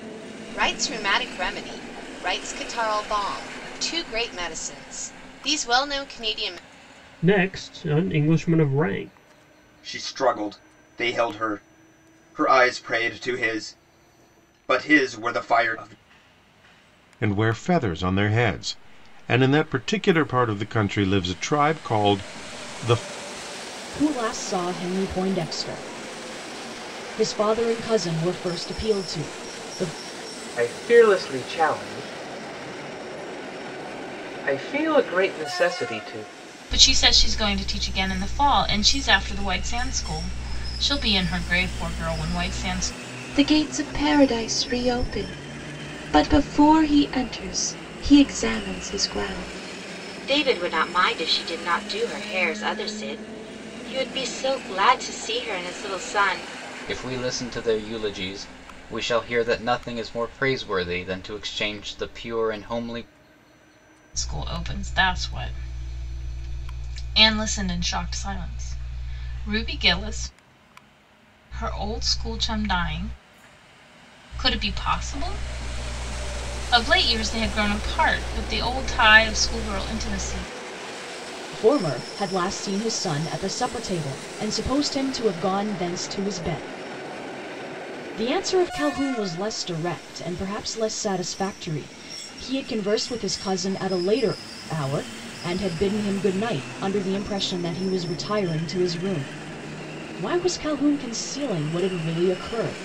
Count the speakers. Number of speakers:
ten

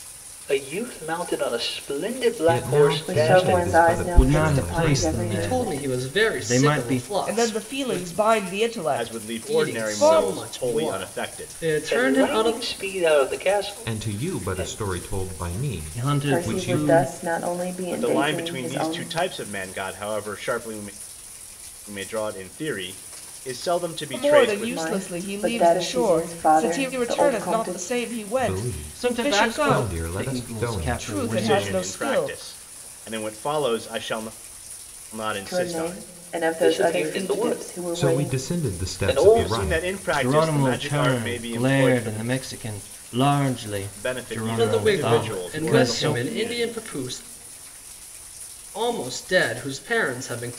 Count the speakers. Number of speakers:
seven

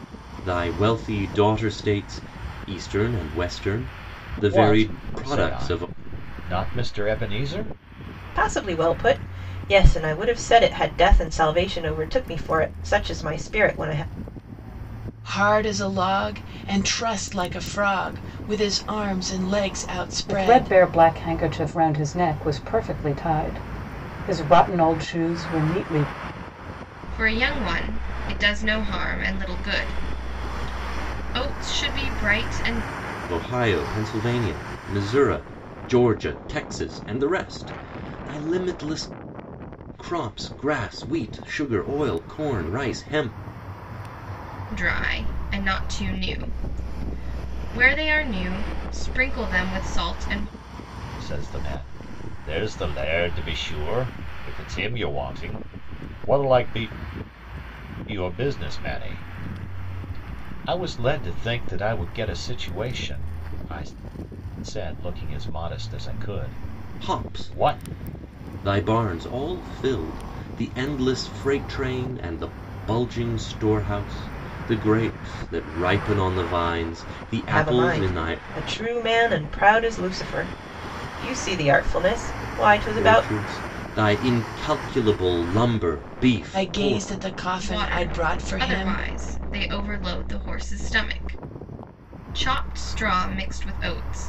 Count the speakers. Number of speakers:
six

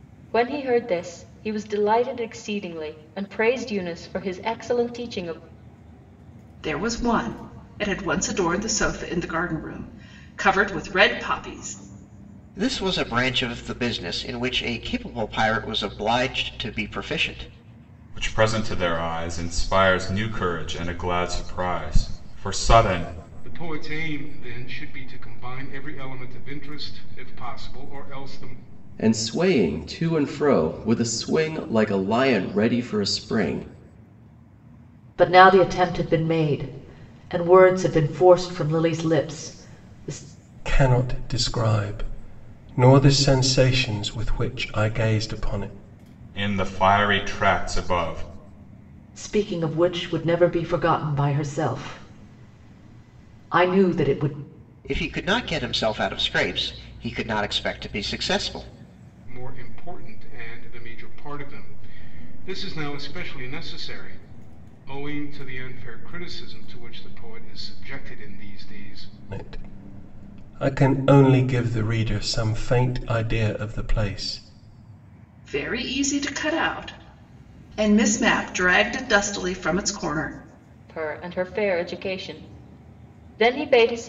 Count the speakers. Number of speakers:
eight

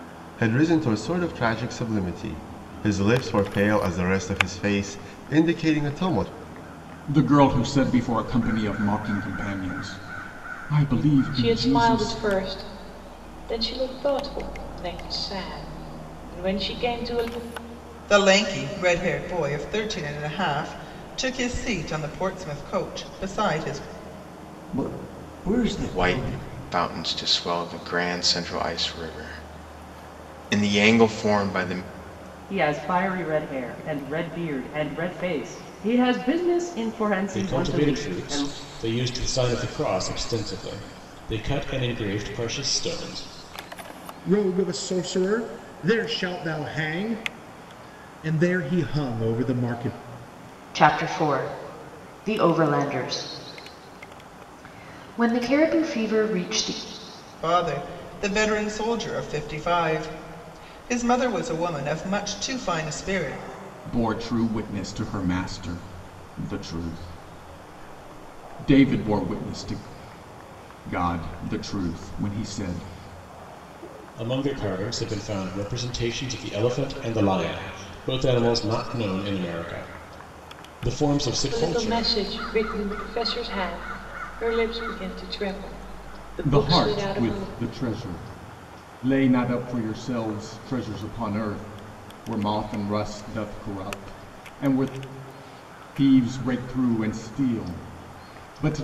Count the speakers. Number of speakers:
ten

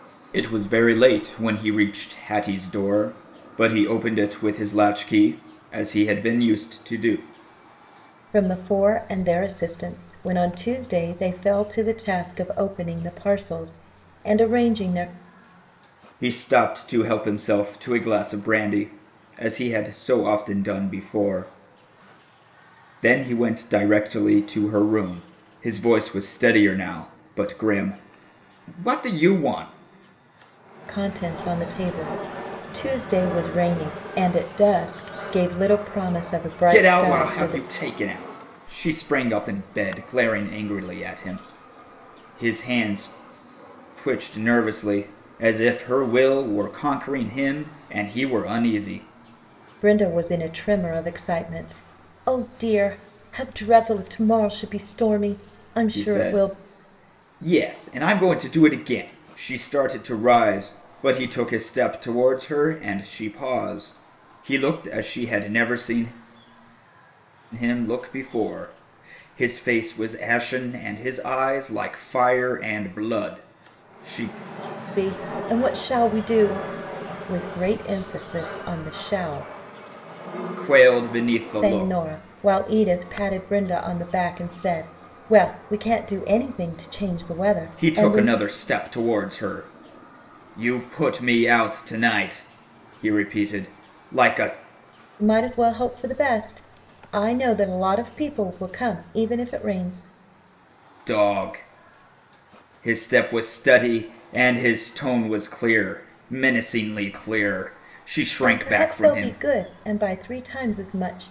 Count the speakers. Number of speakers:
two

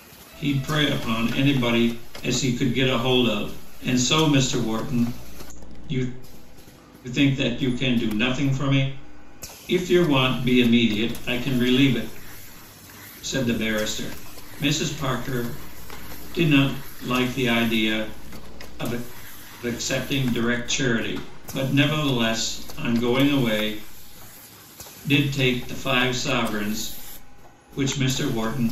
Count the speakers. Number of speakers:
one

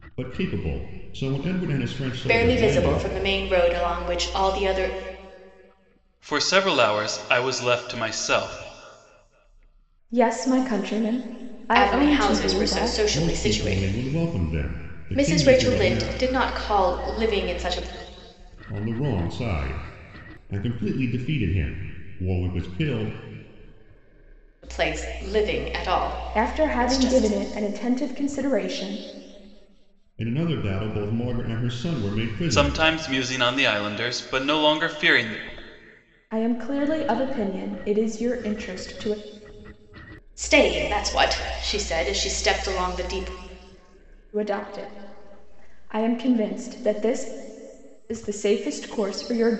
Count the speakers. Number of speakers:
four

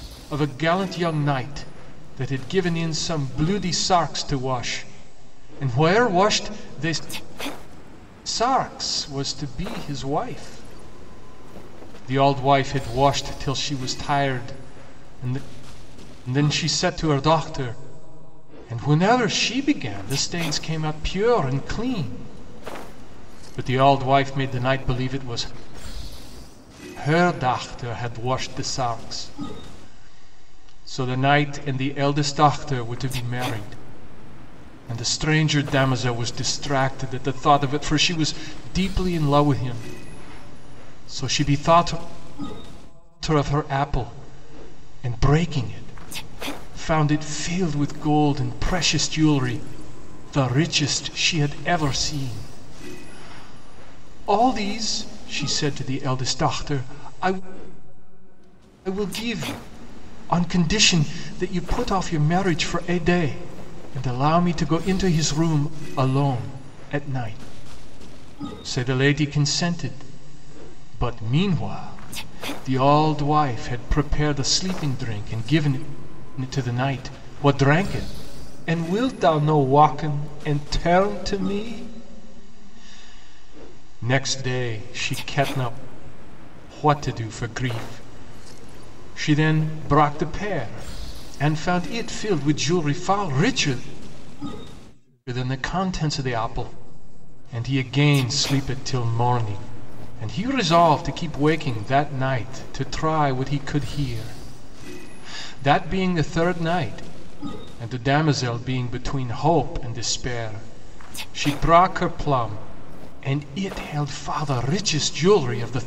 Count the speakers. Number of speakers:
one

